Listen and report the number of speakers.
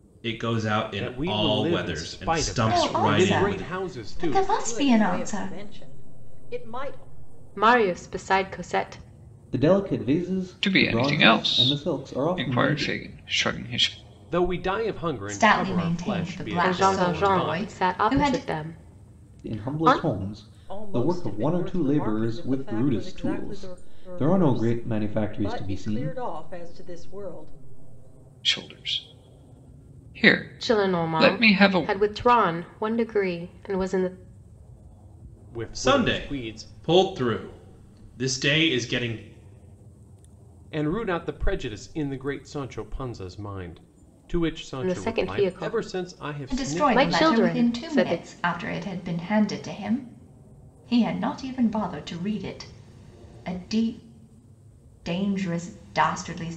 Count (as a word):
seven